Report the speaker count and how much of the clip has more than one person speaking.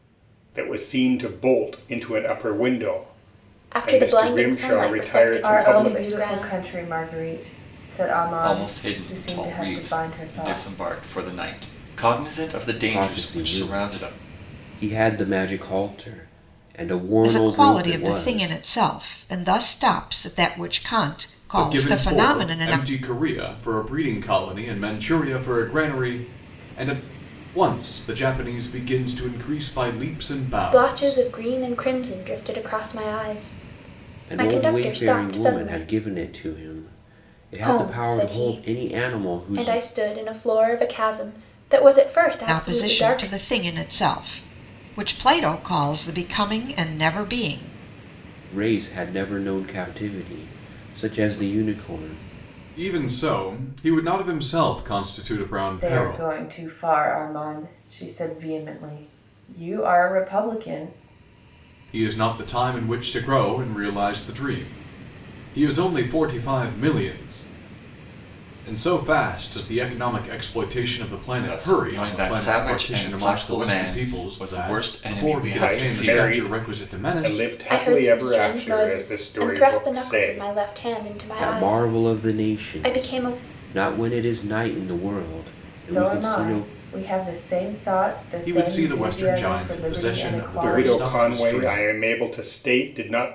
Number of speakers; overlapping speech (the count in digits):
7, about 33%